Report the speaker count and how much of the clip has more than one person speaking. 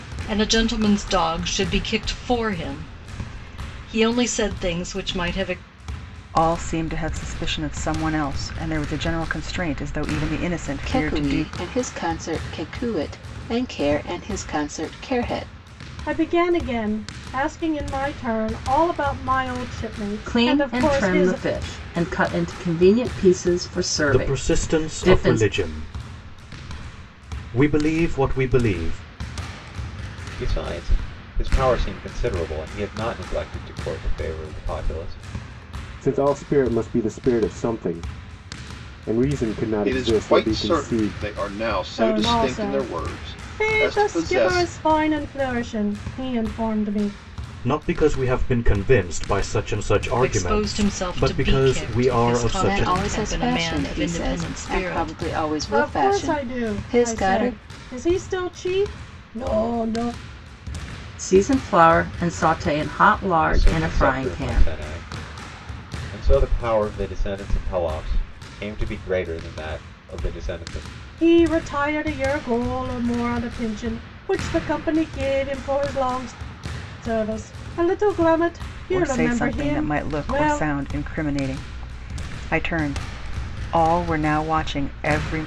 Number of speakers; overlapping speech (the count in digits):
9, about 20%